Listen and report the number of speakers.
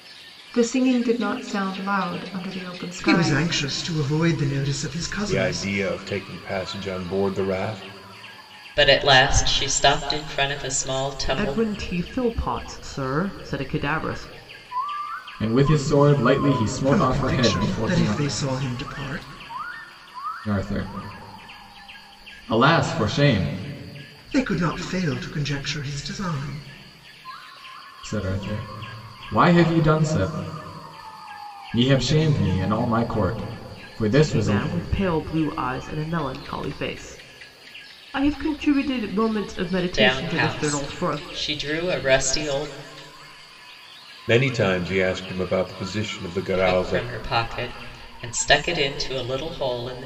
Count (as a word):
six